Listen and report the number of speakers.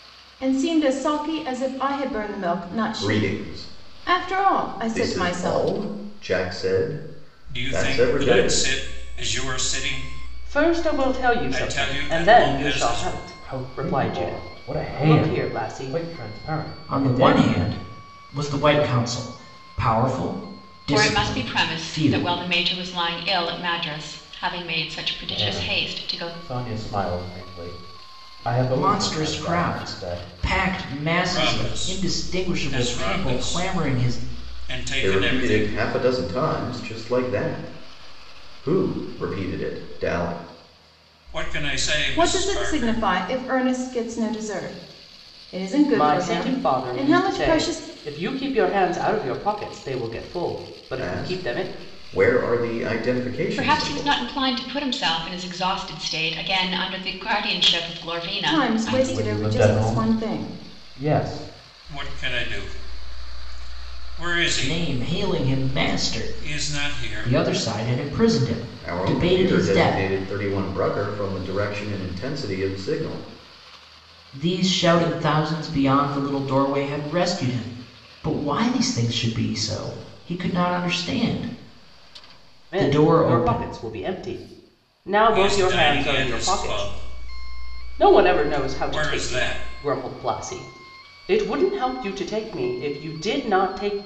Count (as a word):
seven